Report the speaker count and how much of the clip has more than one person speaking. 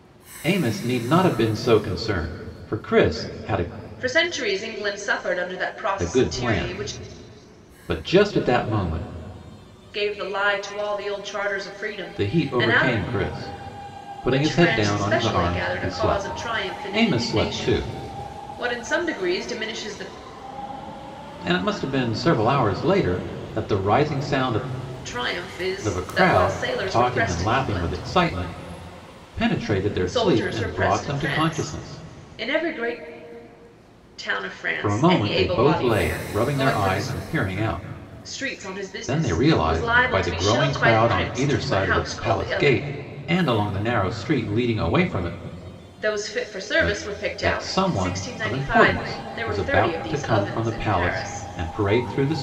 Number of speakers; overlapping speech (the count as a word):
two, about 40%